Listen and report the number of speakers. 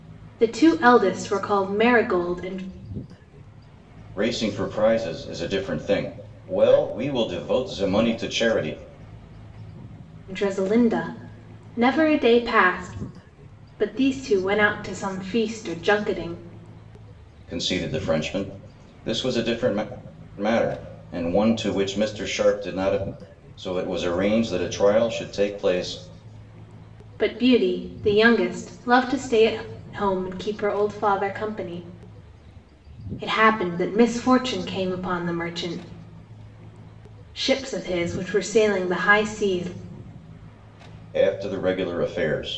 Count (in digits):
2